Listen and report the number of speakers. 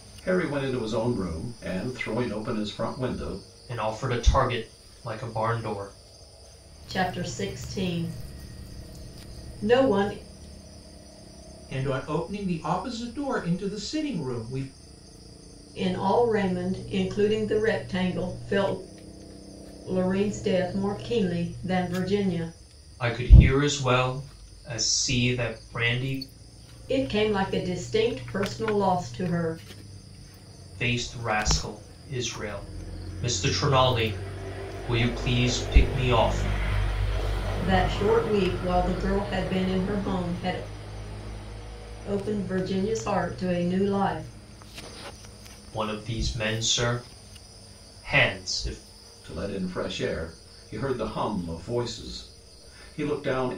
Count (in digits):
4